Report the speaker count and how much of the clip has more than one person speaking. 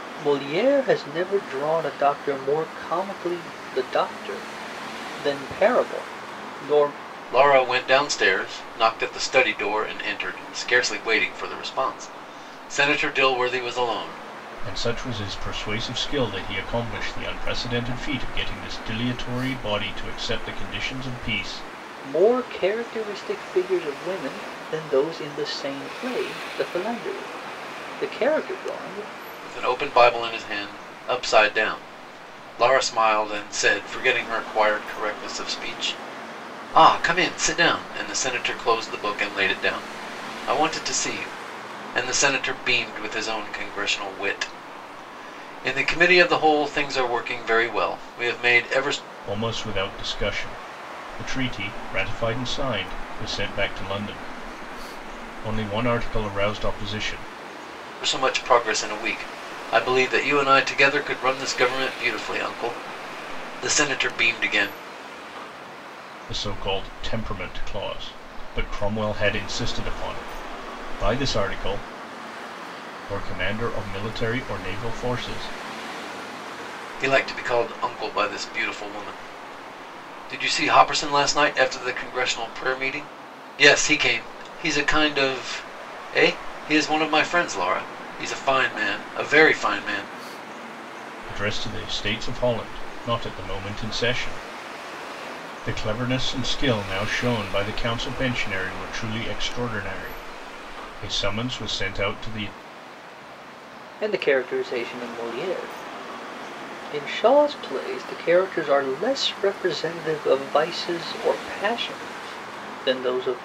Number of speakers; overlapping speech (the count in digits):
3, no overlap